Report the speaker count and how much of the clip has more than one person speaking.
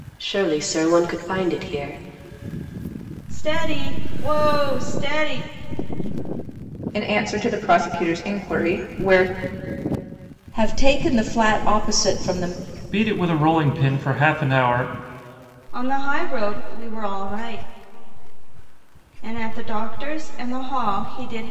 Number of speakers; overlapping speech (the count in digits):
5, no overlap